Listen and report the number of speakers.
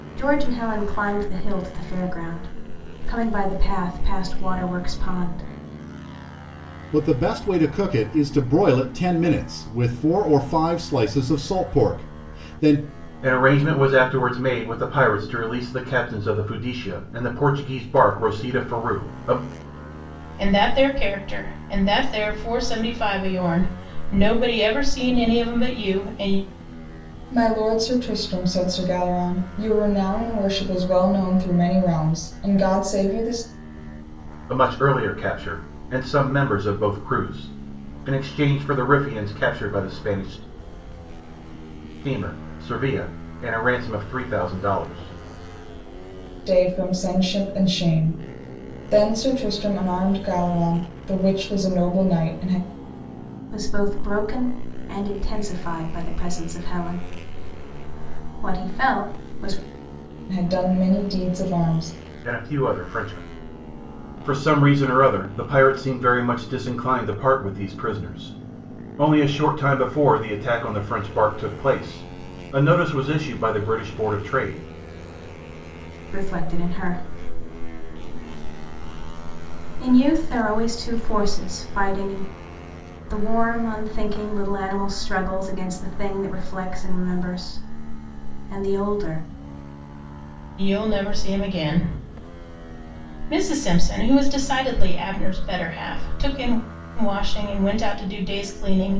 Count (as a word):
five